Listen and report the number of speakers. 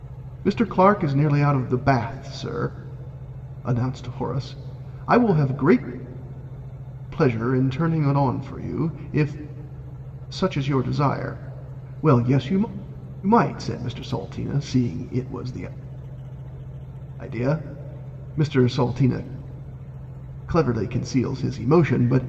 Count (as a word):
one